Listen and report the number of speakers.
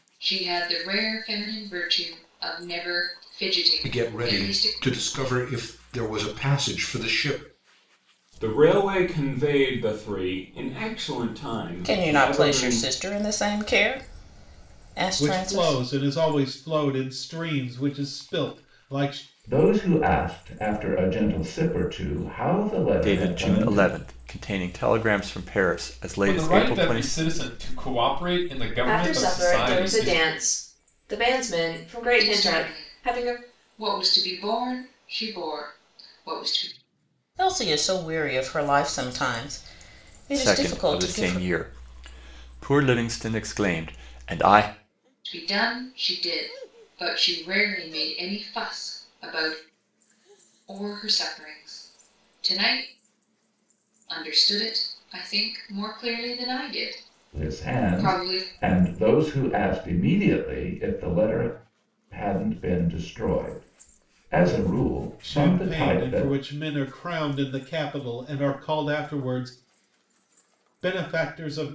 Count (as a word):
nine